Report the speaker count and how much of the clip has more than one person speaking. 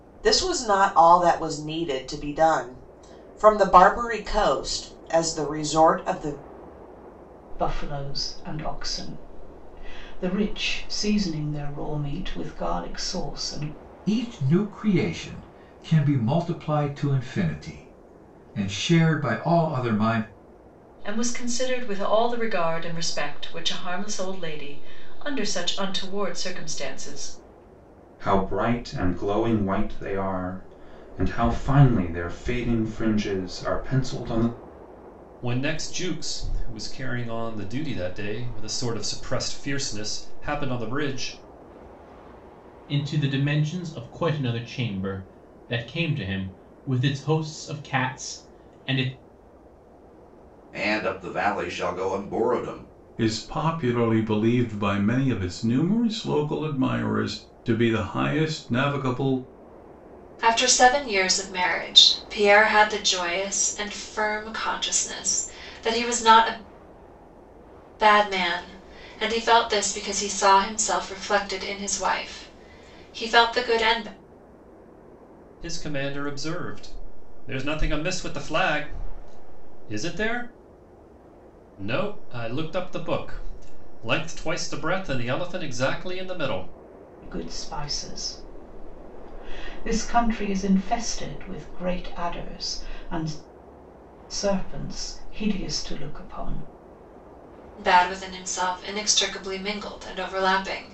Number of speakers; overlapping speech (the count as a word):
ten, no overlap